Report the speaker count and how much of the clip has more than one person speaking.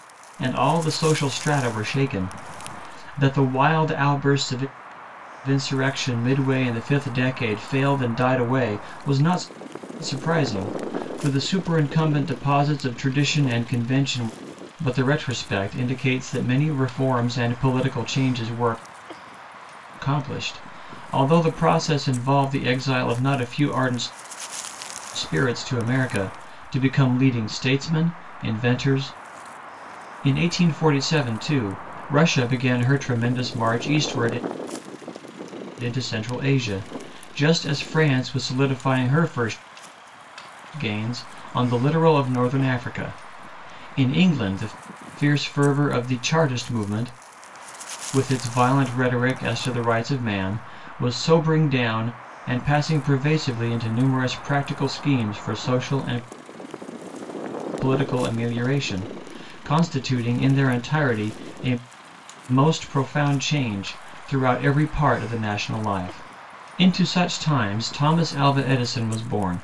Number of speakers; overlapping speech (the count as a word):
one, no overlap